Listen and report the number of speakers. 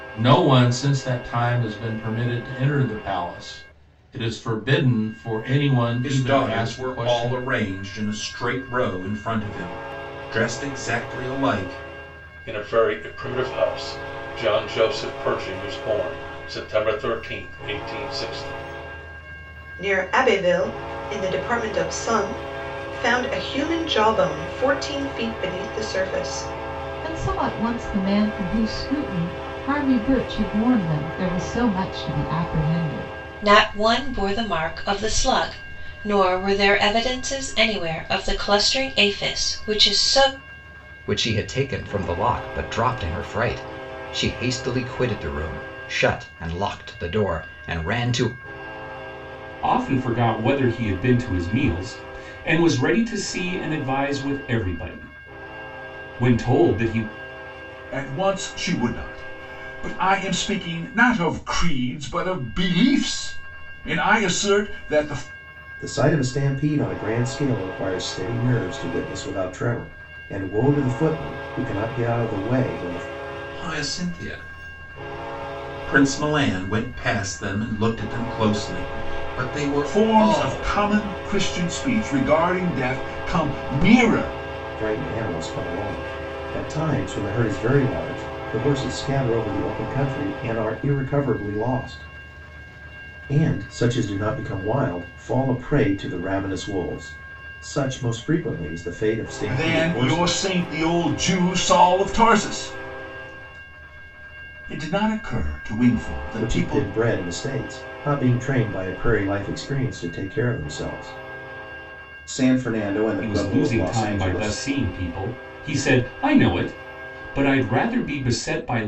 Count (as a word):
ten